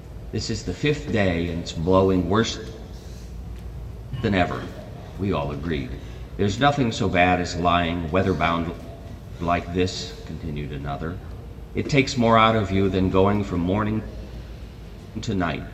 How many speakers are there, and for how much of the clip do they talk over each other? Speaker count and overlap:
1, no overlap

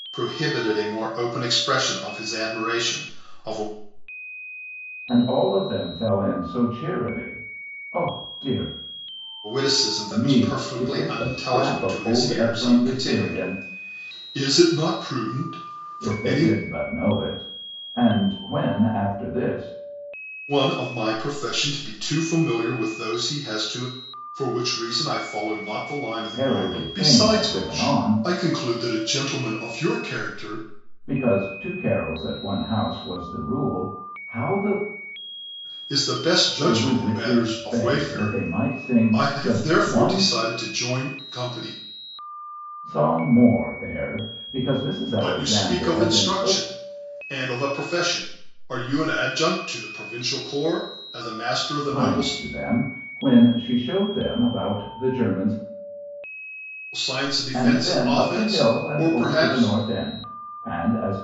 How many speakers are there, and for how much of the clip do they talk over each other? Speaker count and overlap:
2, about 22%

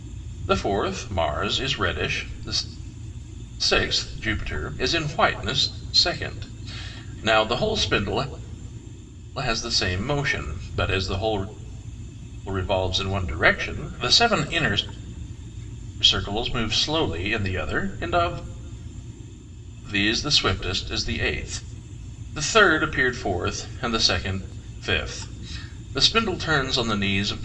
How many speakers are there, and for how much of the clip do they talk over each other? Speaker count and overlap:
1, no overlap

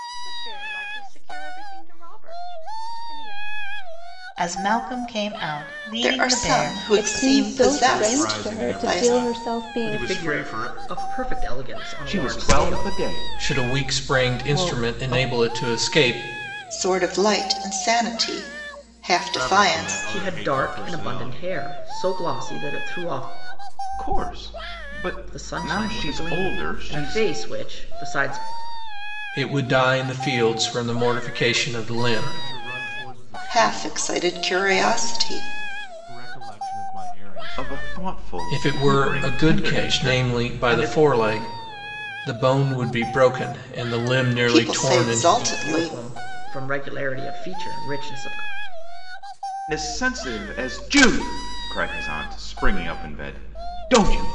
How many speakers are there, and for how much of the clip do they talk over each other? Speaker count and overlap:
8, about 38%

